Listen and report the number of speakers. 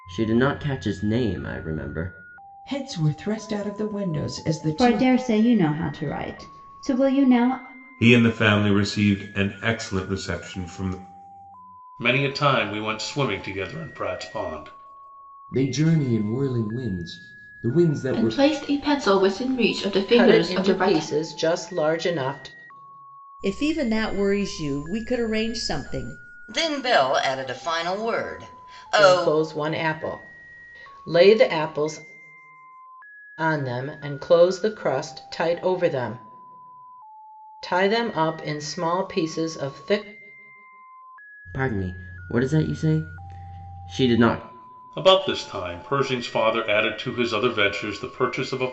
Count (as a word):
ten